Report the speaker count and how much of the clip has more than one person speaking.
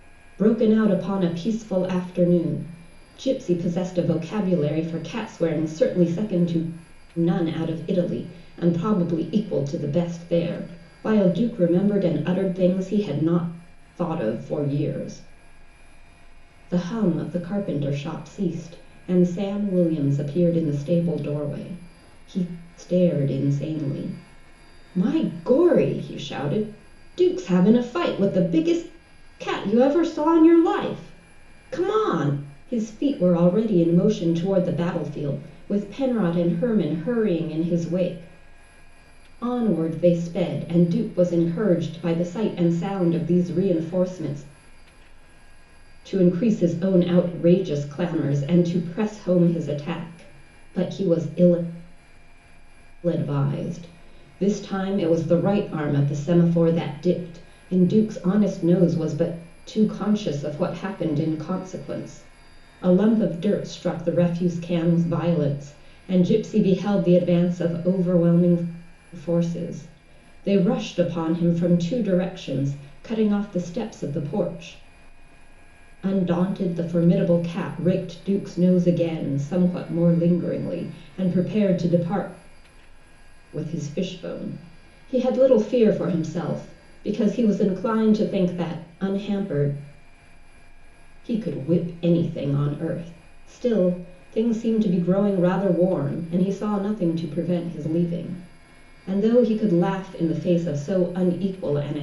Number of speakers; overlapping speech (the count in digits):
1, no overlap